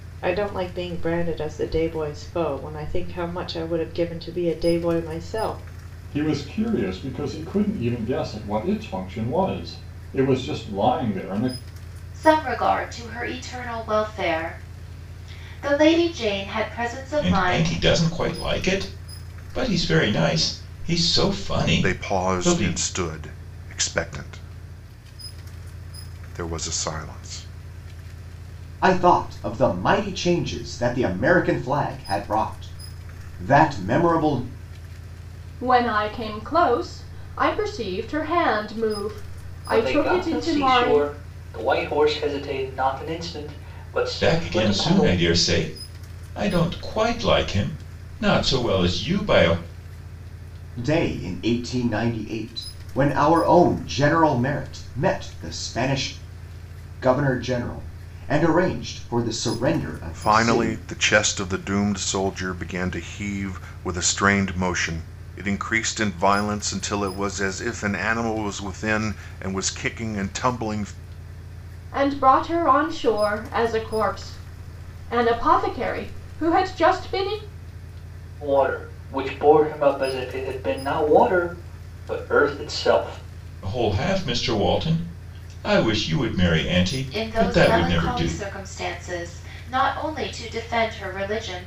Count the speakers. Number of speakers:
eight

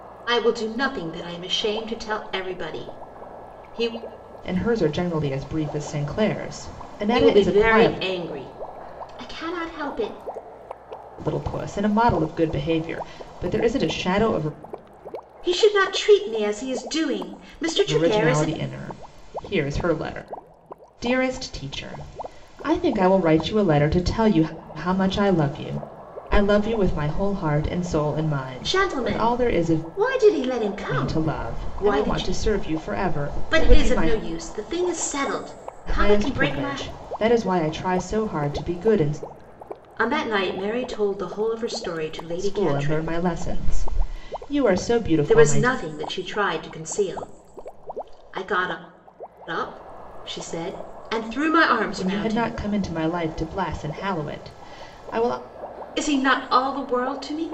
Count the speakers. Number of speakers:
two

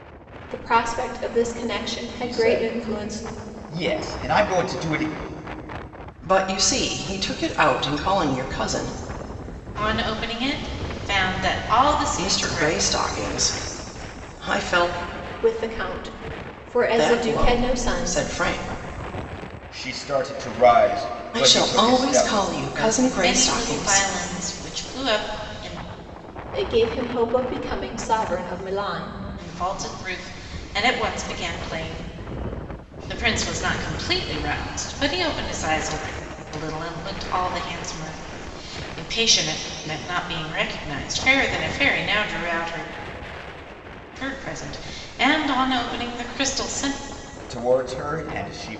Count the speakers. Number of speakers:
four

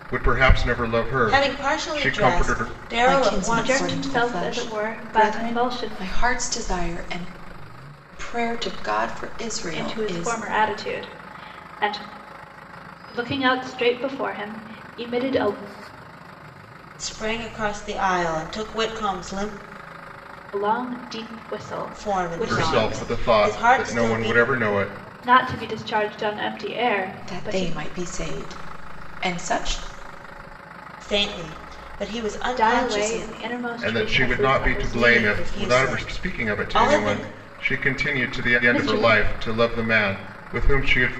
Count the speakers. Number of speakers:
four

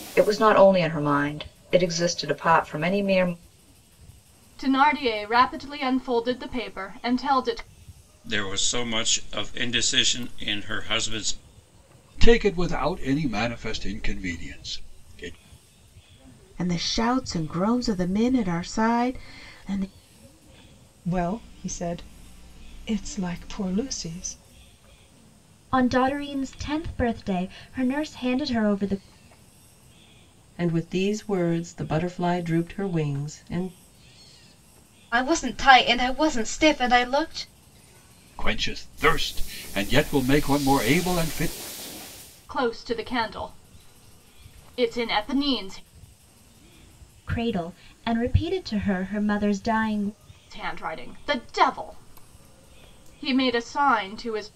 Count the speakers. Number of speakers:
nine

